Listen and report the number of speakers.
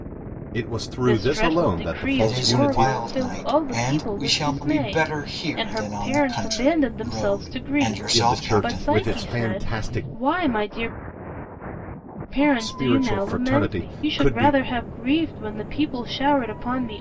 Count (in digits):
3